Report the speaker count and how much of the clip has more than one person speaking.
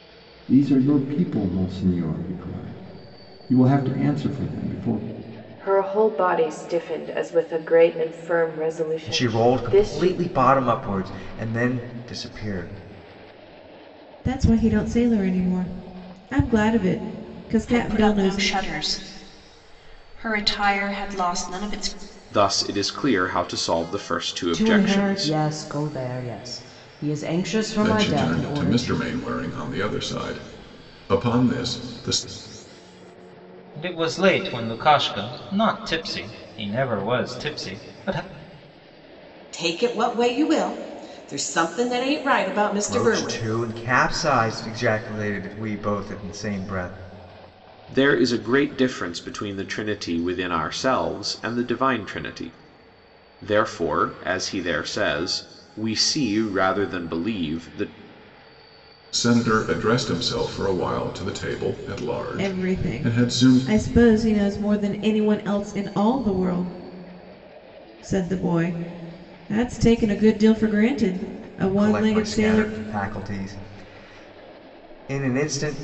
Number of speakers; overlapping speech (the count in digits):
10, about 9%